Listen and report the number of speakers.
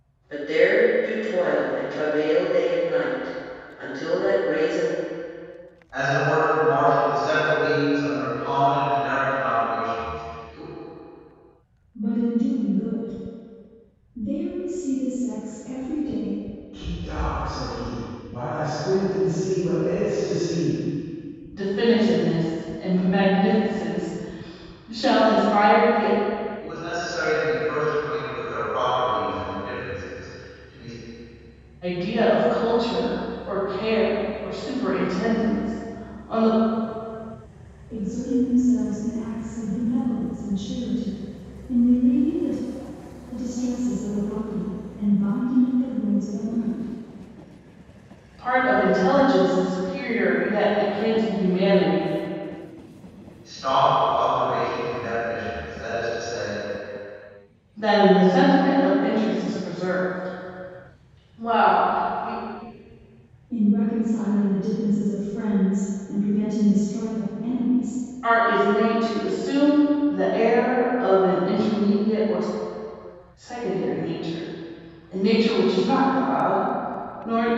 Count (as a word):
five